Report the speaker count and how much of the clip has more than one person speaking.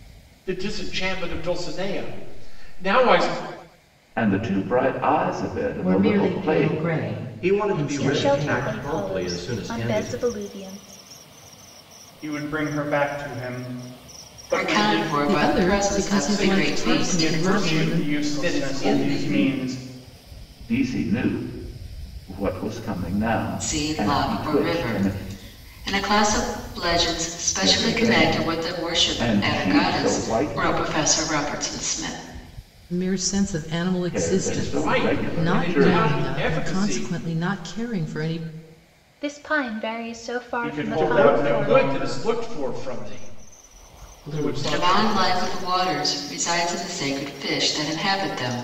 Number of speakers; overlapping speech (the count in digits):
8, about 40%